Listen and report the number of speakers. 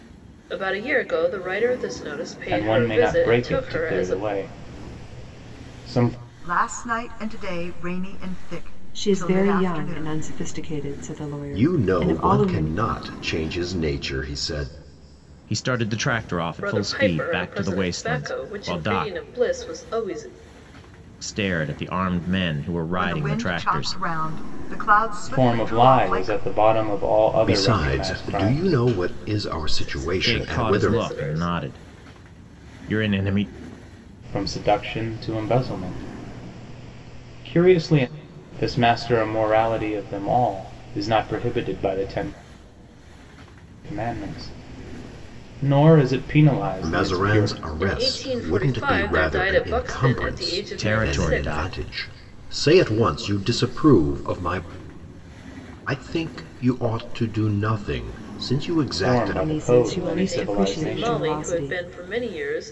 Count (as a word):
six